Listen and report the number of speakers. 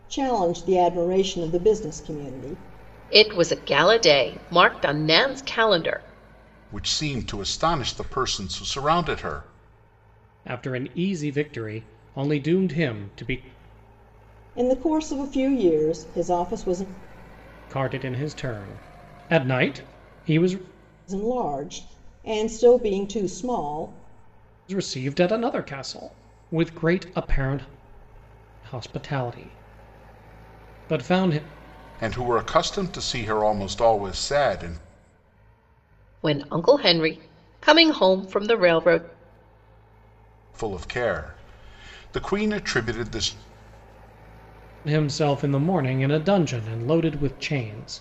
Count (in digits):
4